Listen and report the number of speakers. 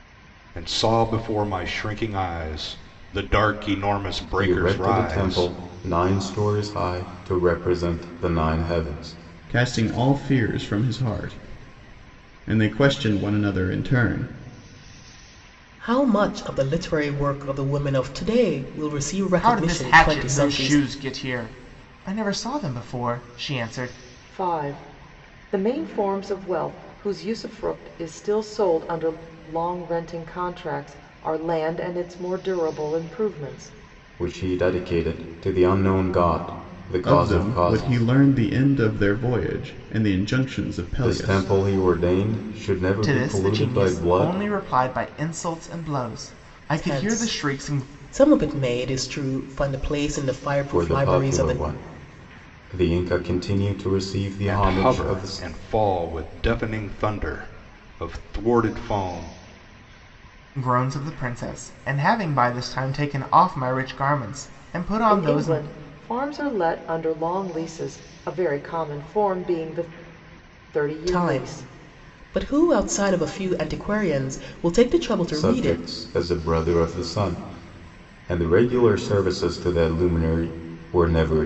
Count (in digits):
6